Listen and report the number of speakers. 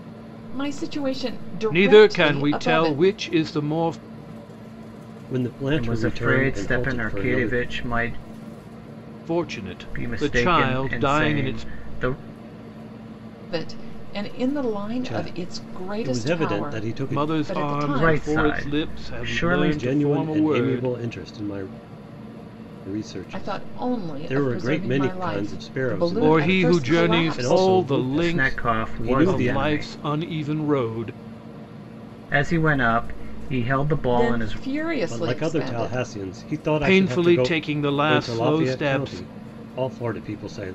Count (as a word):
four